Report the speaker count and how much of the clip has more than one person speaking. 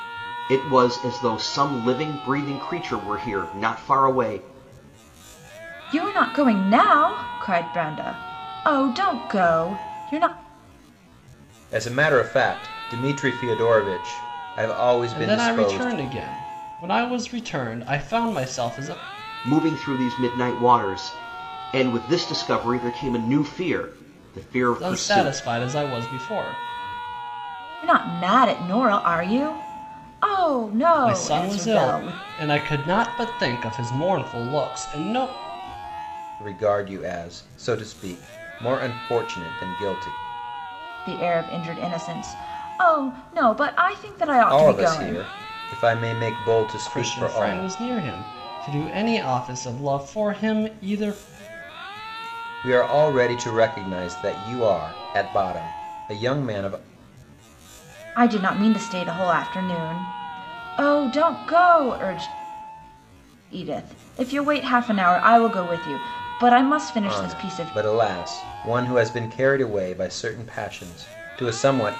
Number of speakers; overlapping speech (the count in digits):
4, about 8%